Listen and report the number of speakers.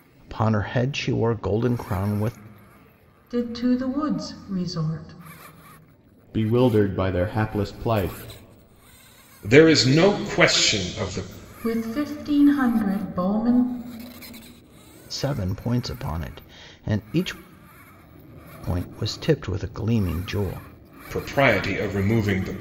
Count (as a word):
four